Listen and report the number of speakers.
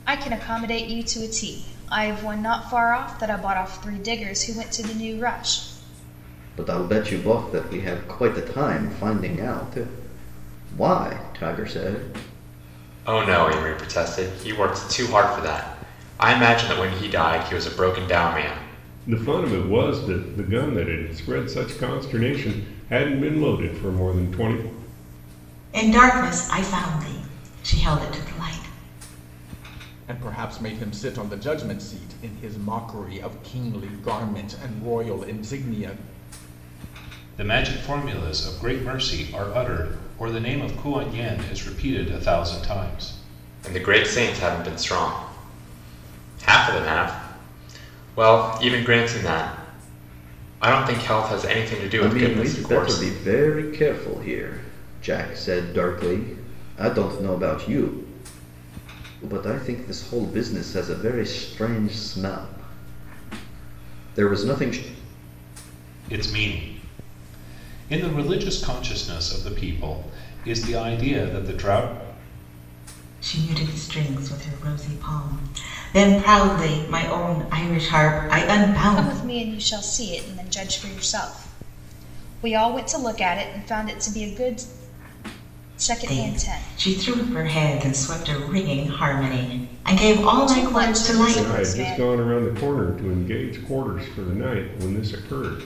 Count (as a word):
seven